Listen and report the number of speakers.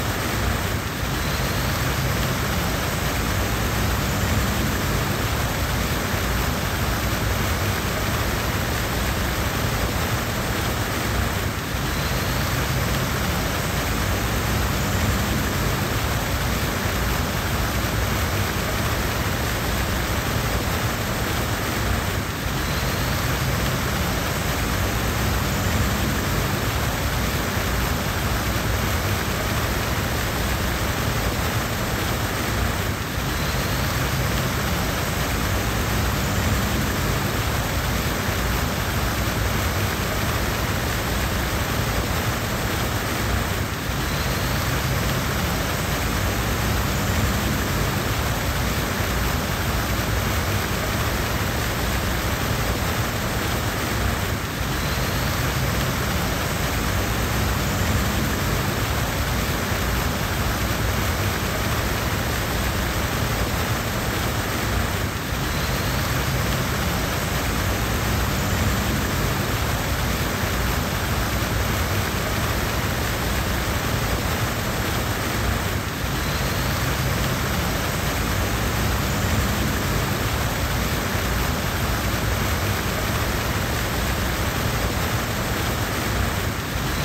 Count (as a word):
zero